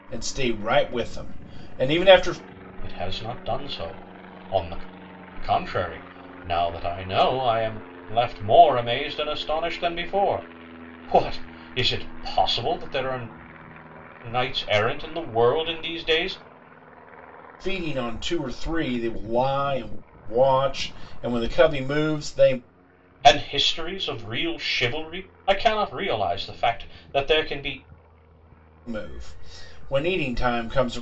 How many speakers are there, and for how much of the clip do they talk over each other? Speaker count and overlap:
2, no overlap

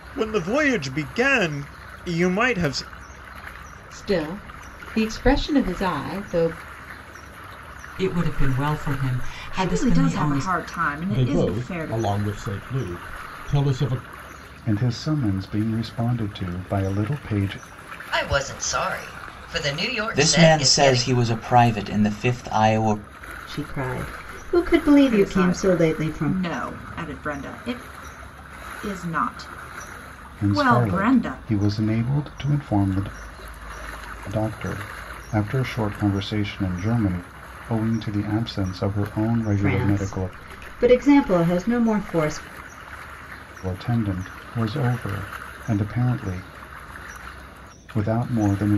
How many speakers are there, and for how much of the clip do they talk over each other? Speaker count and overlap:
9, about 13%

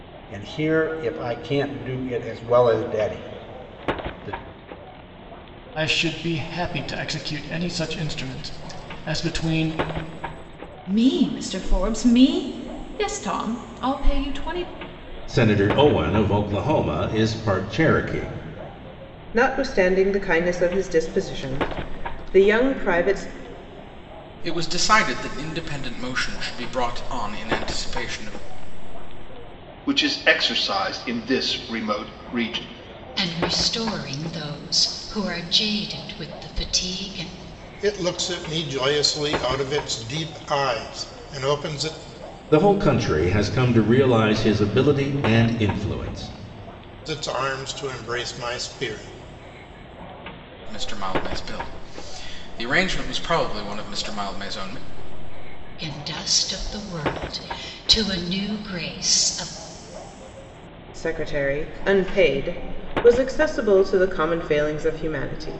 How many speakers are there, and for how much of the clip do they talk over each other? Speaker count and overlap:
9, no overlap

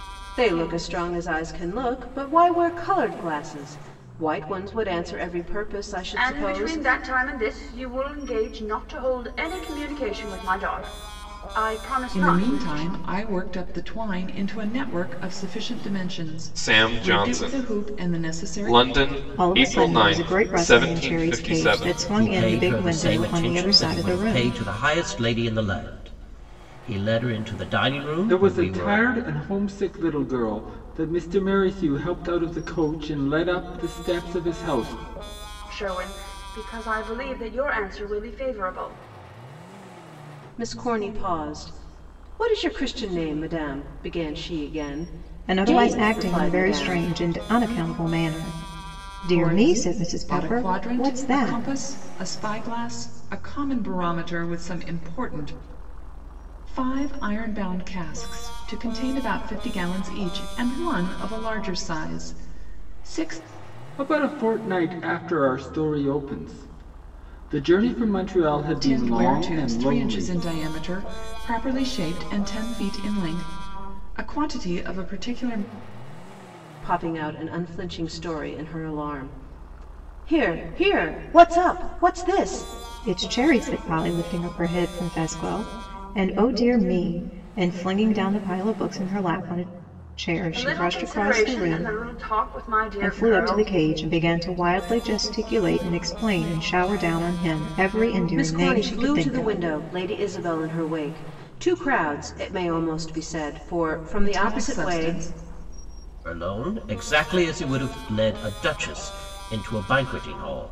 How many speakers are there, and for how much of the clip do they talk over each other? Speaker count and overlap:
7, about 18%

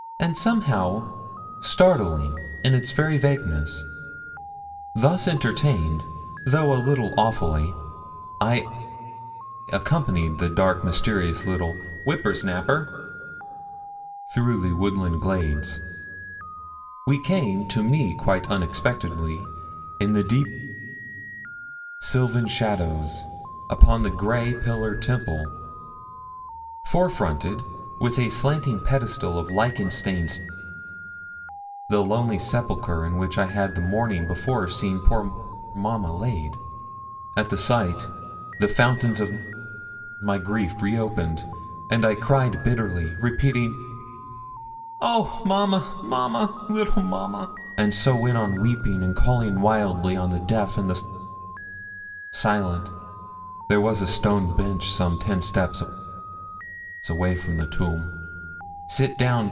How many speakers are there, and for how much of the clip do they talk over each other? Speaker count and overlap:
1, no overlap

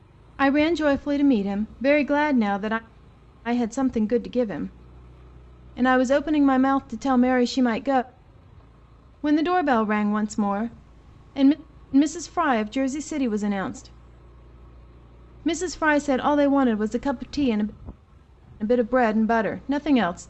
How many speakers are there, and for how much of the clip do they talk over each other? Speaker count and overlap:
1, no overlap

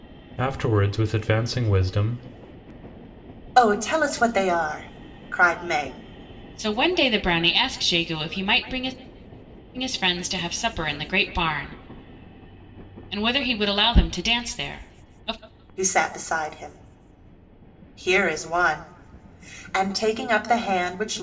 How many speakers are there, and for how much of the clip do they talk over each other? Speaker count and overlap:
3, no overlap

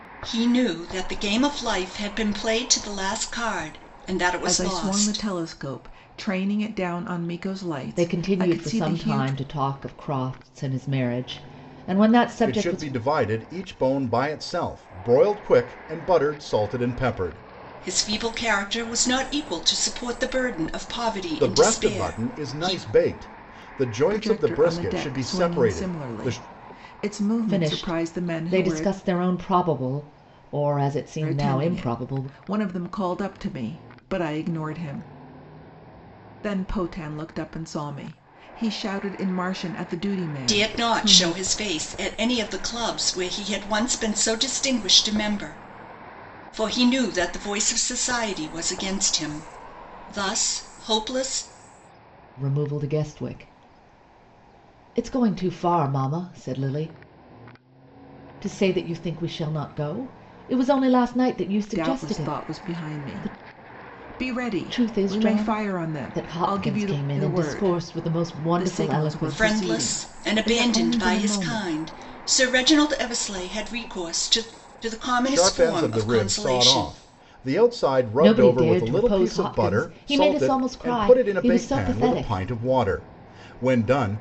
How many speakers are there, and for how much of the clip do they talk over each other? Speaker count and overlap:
4, about 29%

